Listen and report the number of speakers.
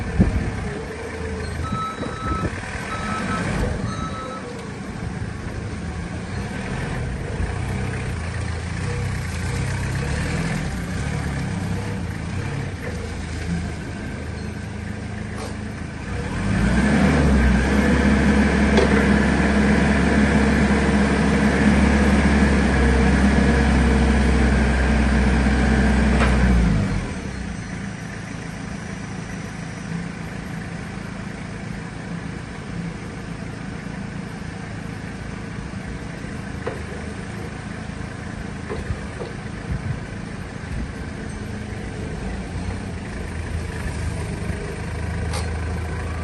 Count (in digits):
0